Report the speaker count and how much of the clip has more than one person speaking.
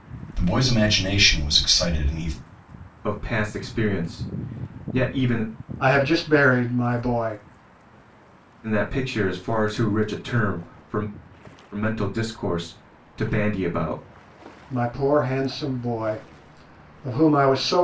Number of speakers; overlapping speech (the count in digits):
3, no overlap